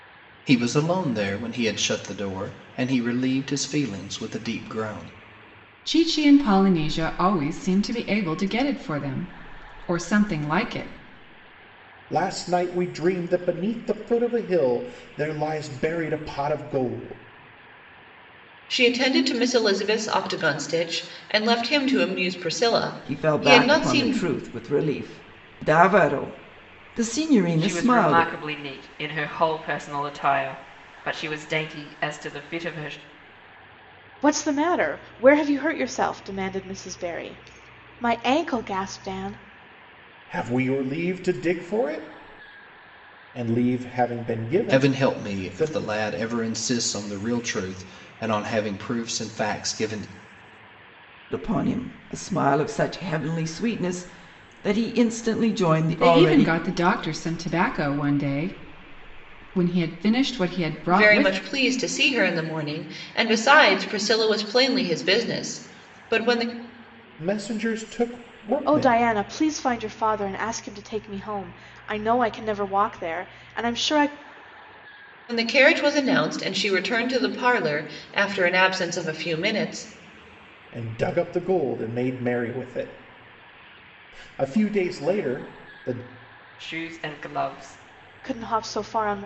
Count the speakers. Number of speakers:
7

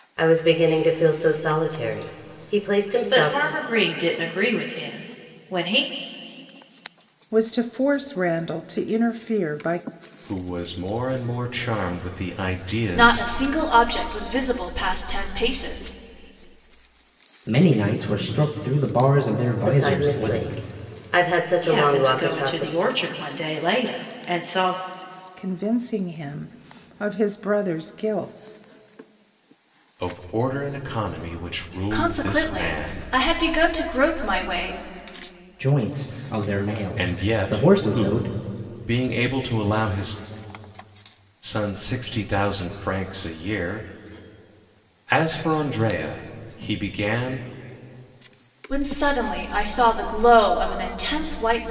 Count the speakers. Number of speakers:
6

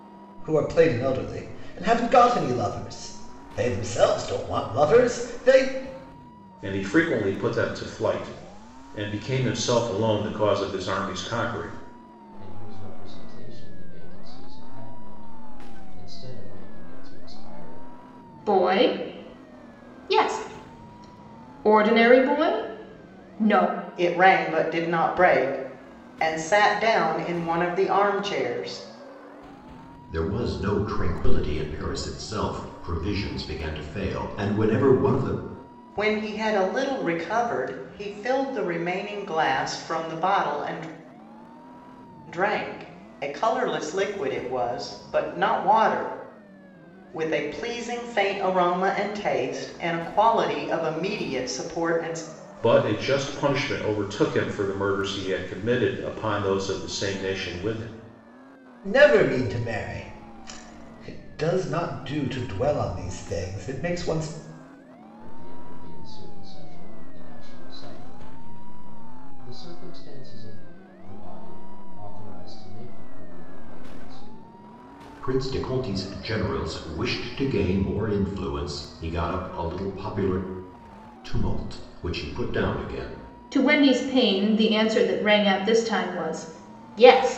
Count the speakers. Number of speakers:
6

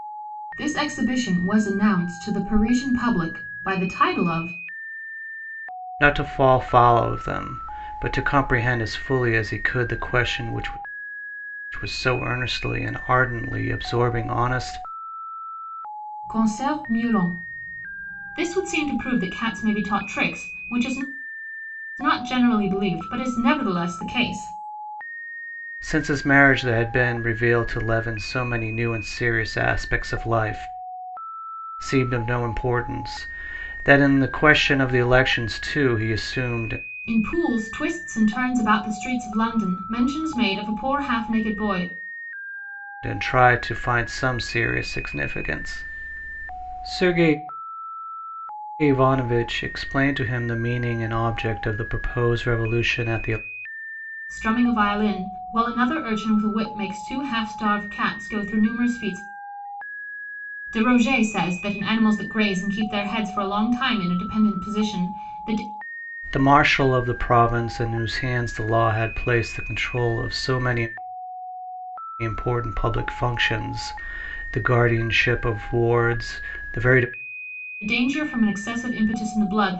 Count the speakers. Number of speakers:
2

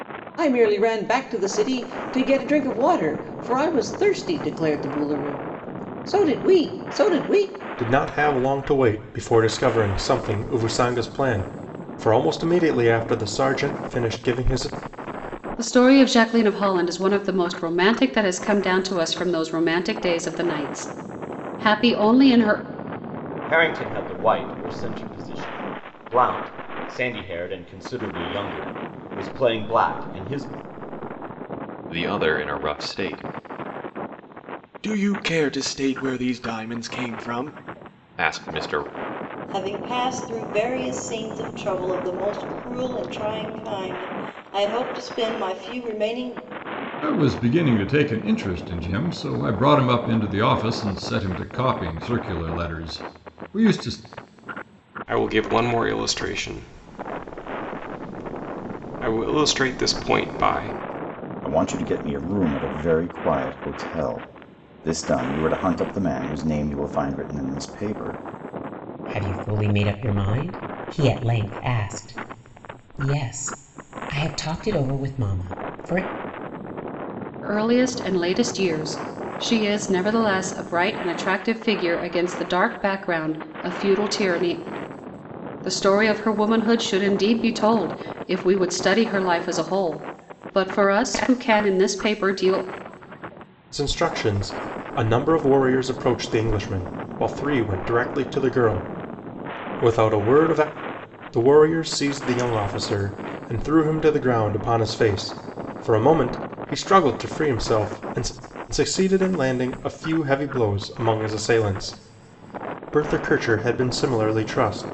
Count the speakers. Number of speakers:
10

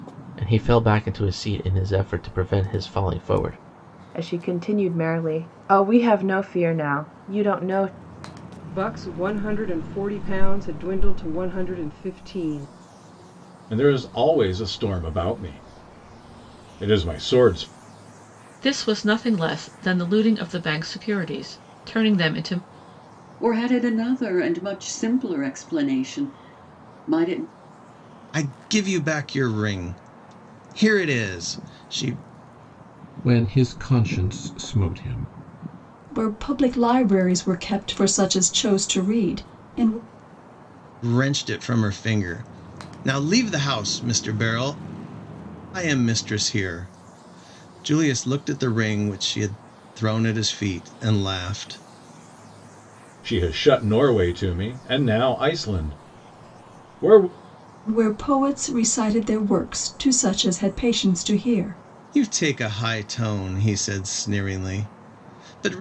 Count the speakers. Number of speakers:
9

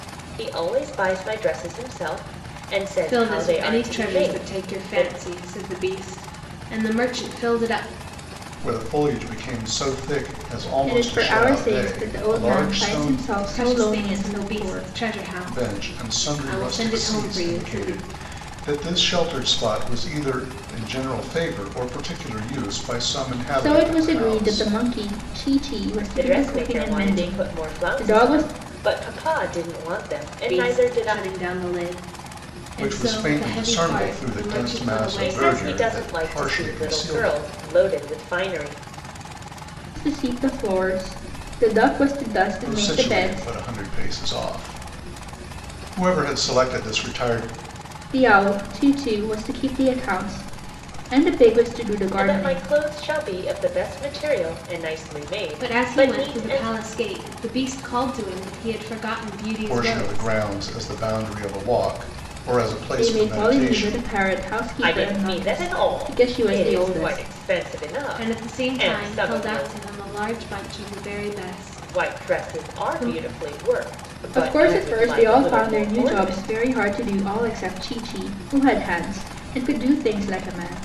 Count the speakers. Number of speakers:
4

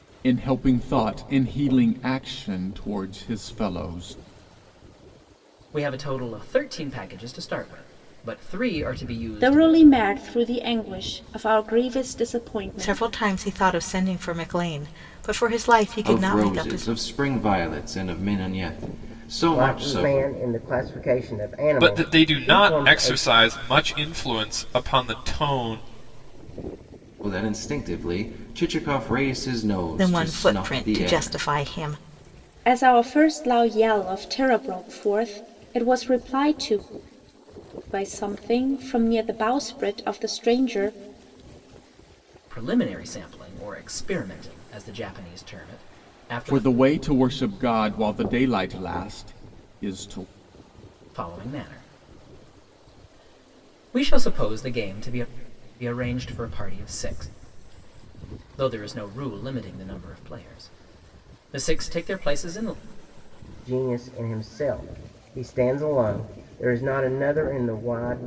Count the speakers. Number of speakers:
7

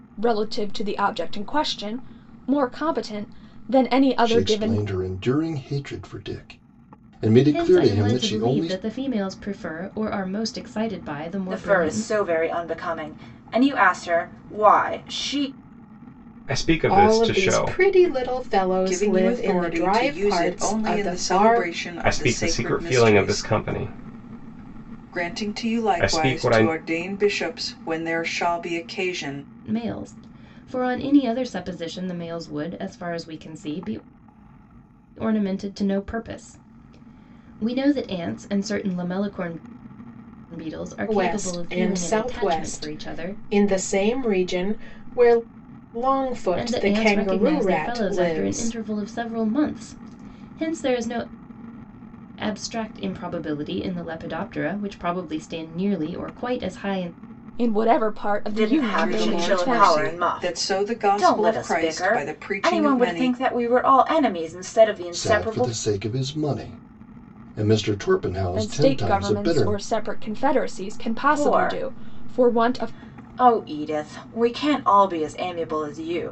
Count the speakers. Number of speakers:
7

